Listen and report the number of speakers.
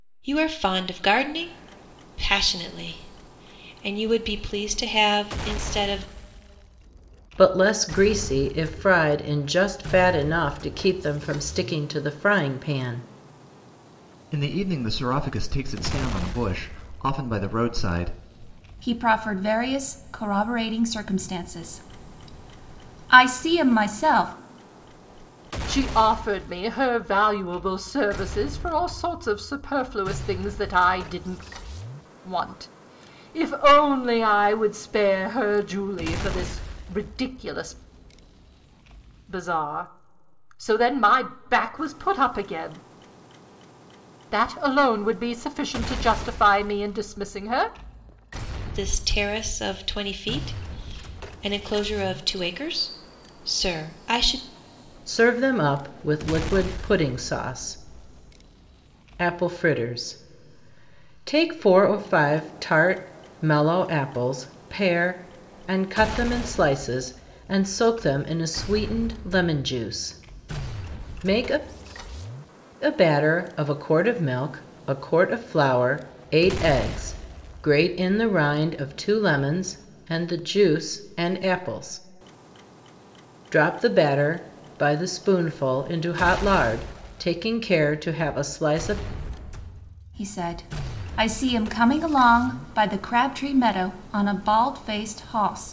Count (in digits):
5